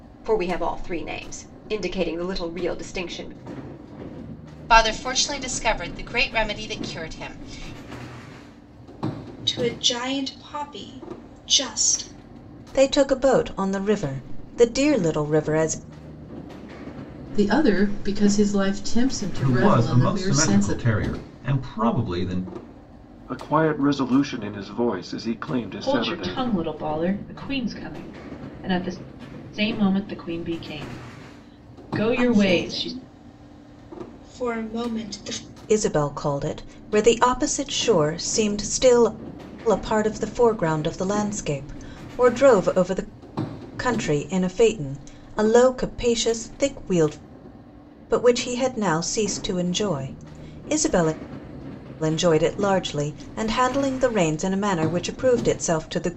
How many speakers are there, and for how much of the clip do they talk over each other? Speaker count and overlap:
8, about 5%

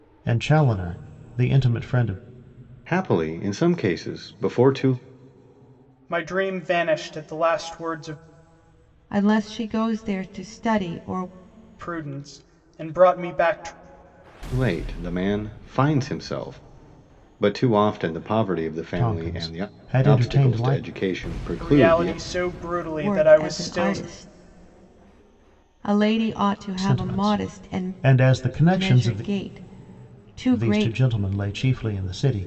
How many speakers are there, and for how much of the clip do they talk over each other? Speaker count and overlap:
4, about 17%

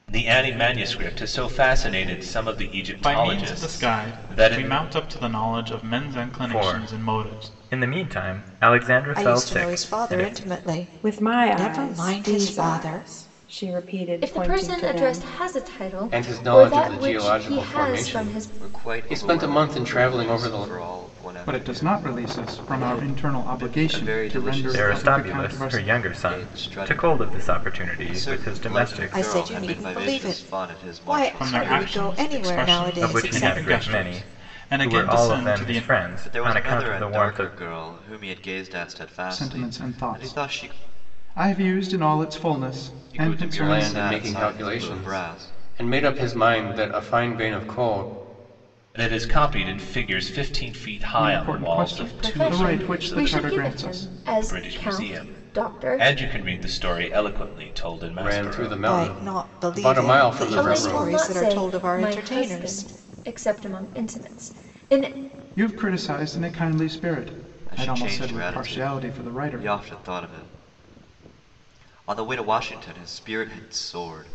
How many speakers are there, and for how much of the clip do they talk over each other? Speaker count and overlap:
9, about 56%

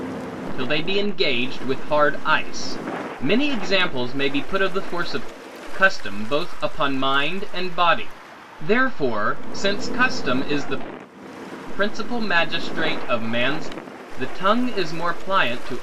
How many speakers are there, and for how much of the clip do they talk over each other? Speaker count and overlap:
1, no overlap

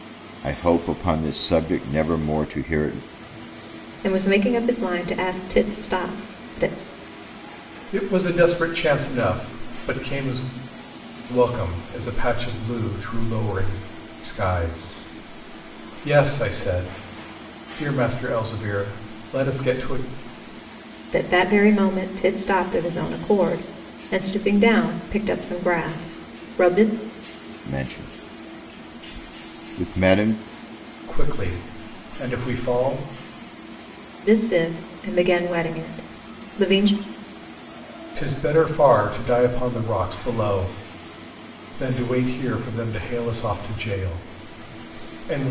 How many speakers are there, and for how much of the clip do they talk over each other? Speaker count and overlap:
3, no overlap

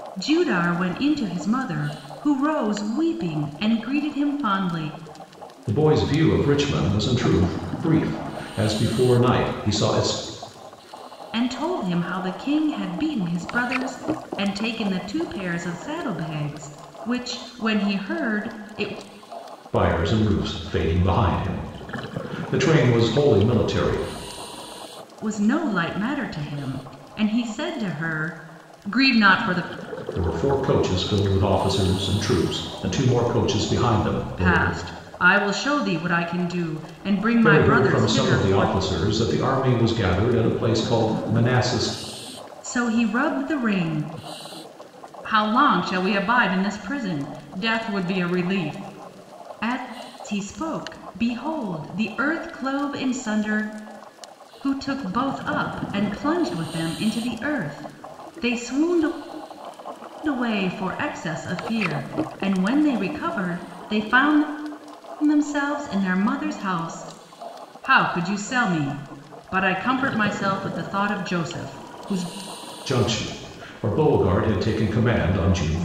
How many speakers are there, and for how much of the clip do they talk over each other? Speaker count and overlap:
2, about 3%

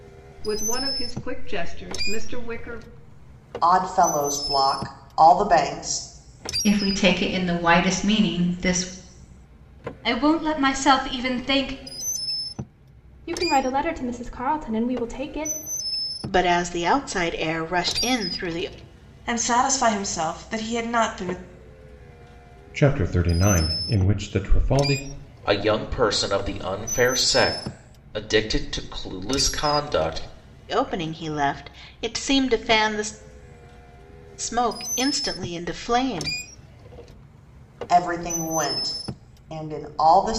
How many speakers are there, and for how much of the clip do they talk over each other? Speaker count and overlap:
9, no overlap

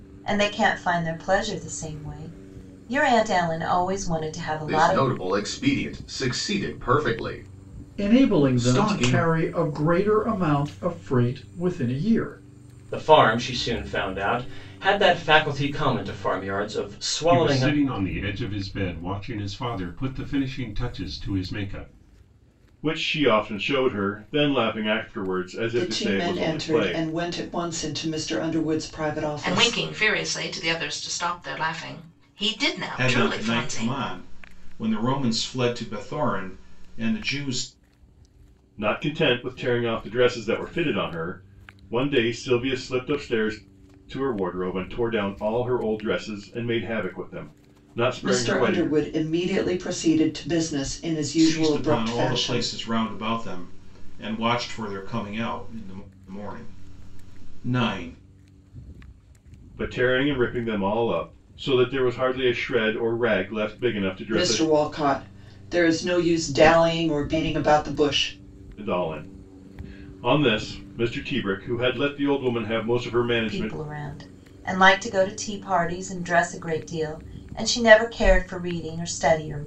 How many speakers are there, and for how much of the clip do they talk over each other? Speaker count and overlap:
9, about 10%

